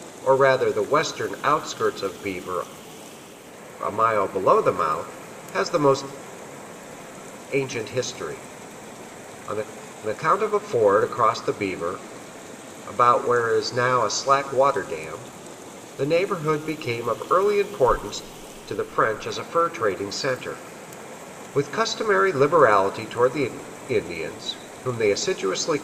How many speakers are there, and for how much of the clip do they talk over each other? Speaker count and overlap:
1, no overlap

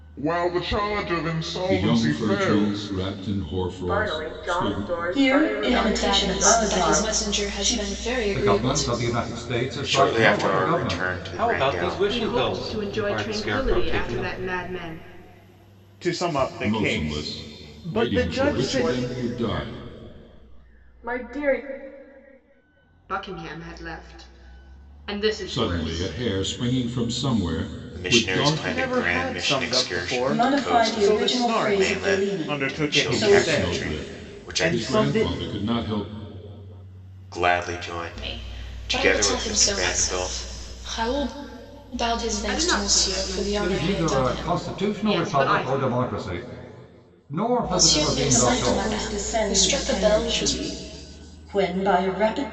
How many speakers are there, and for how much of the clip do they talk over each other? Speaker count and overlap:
9, about 57%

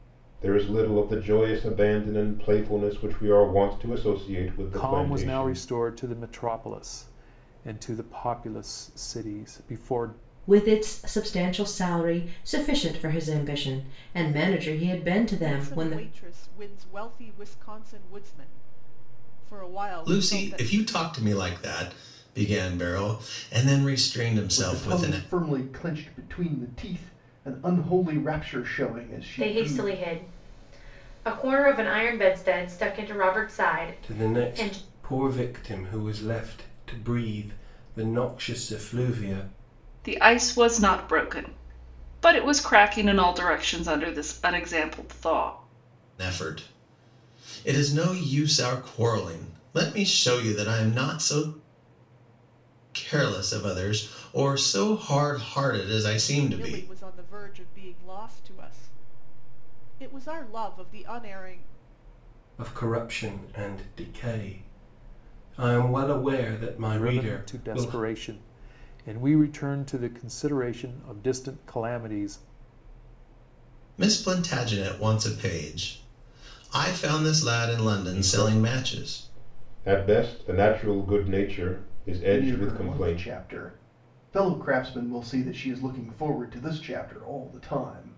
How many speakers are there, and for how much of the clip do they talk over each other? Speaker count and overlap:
9, about 9%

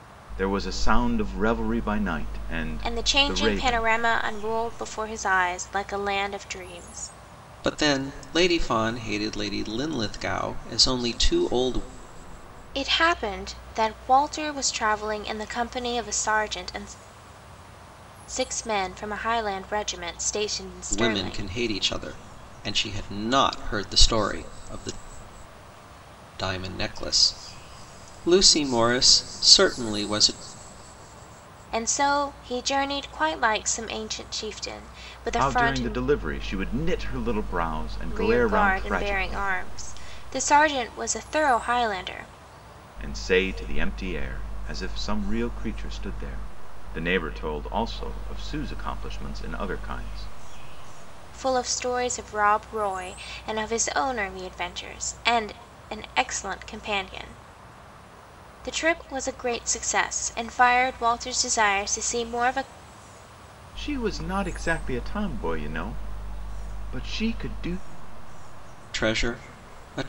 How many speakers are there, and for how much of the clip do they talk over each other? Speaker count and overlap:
3, about 5%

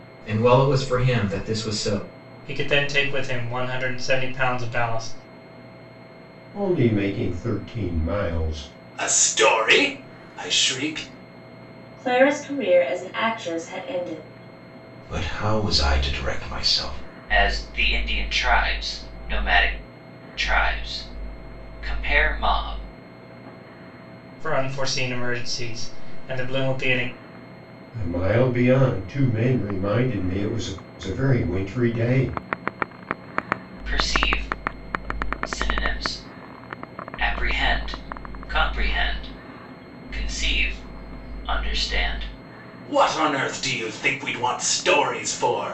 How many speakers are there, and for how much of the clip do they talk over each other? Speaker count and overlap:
7, no overlap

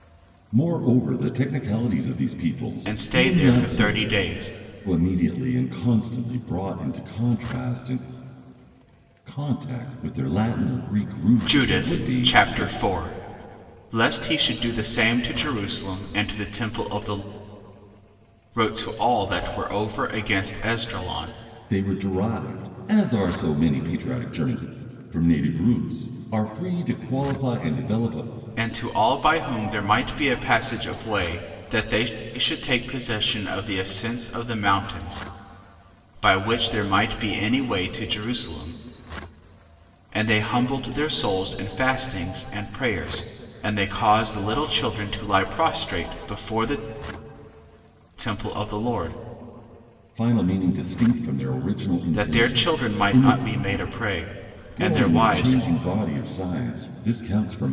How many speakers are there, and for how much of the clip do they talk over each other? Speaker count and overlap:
2, about 8%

